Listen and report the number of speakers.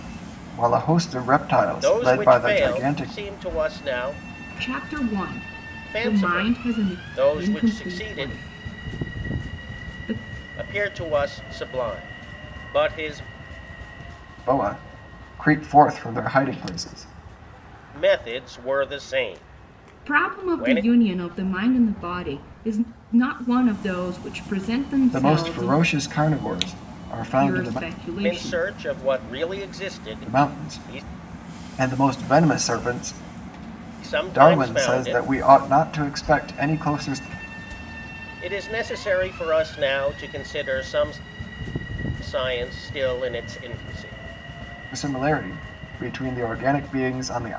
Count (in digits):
3